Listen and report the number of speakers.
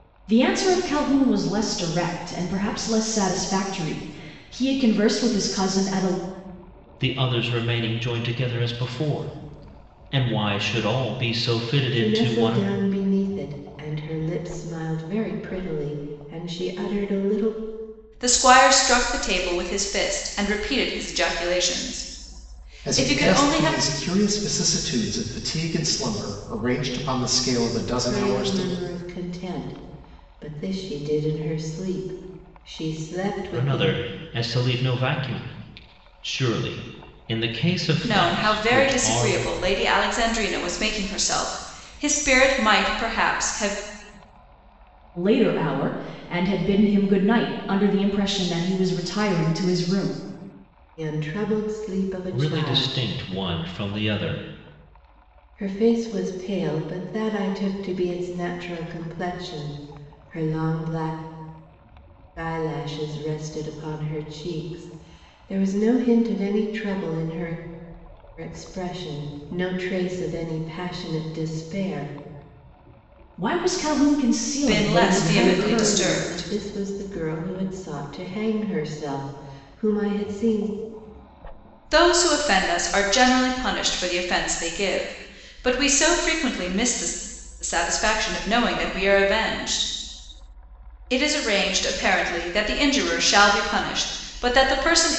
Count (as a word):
five